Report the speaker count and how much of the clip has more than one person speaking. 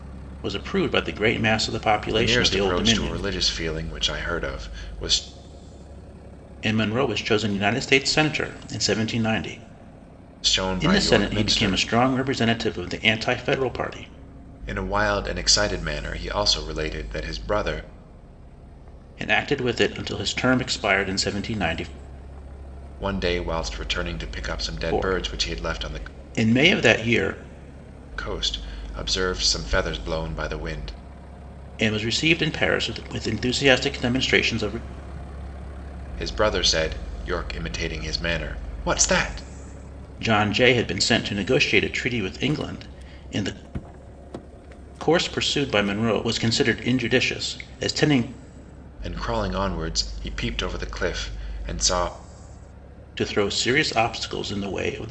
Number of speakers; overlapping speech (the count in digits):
2, about 6%